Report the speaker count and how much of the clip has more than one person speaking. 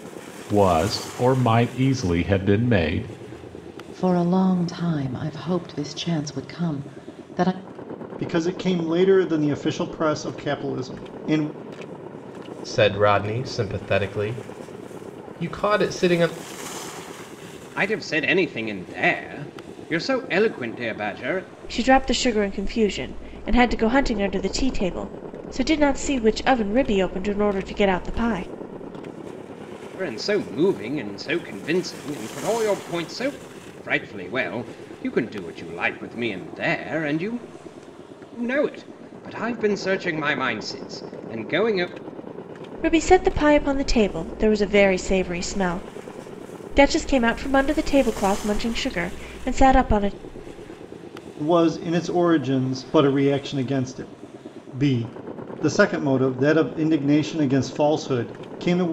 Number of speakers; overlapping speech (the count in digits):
6, no overlap